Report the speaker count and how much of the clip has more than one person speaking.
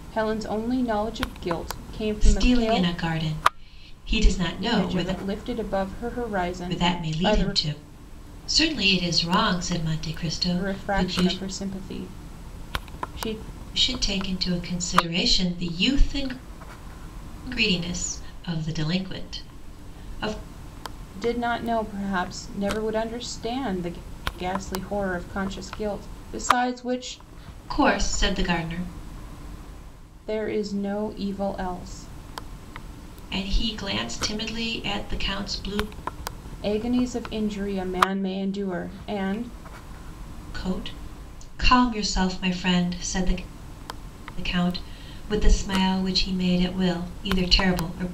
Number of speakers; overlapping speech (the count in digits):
2, about 6%